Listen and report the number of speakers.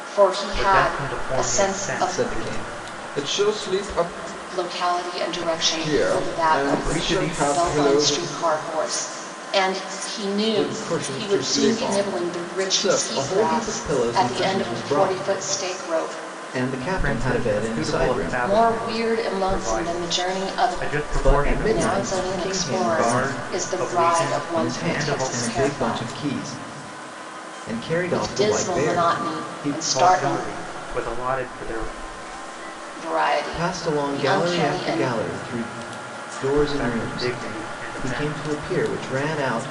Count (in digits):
3